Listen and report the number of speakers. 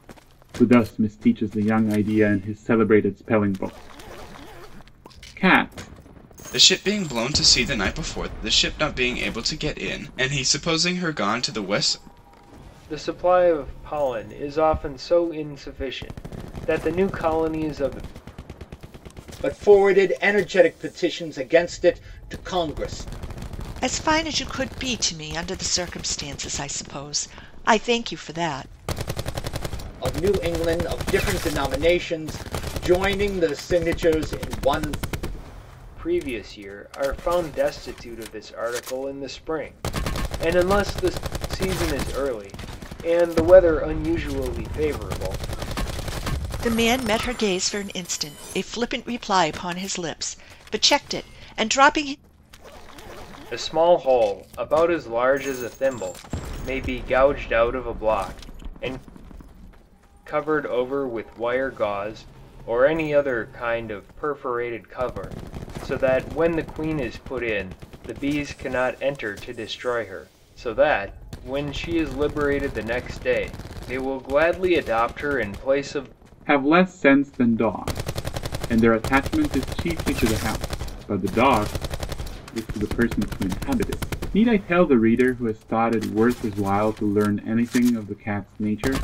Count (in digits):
5